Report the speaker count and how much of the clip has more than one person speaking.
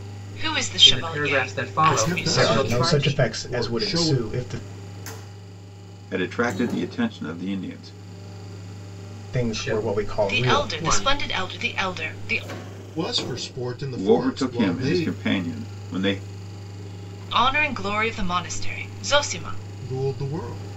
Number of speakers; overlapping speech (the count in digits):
5, about 30%